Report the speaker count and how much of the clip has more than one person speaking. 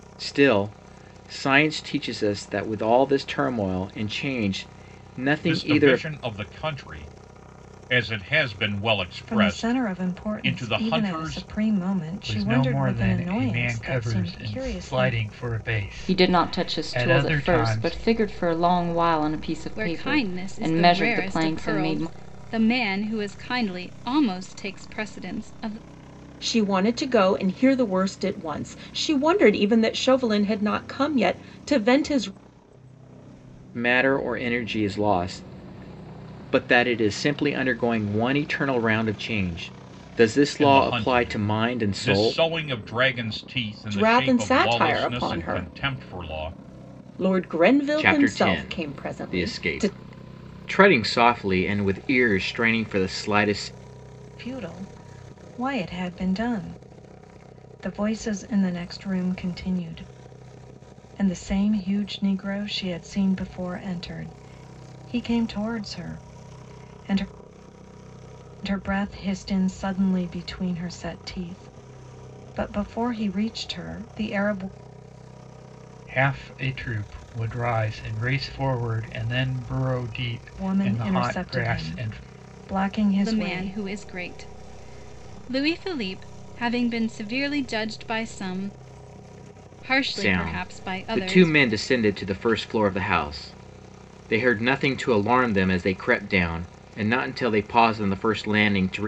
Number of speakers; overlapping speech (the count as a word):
seven, about 21%